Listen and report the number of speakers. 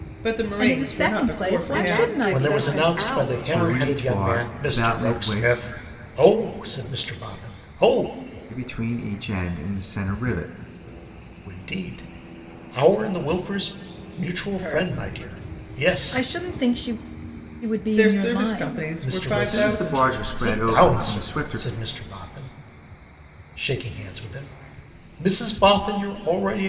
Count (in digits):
5